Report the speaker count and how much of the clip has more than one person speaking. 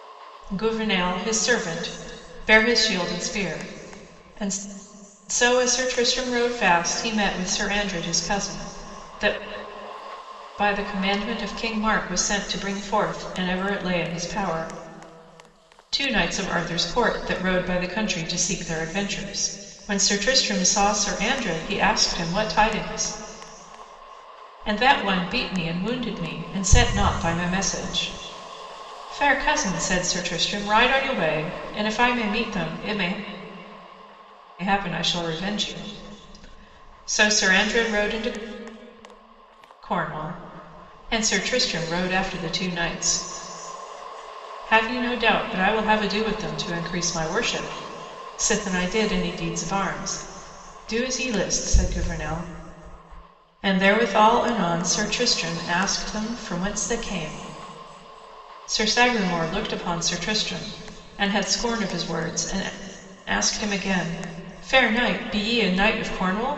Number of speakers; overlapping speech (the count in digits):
1, no overlap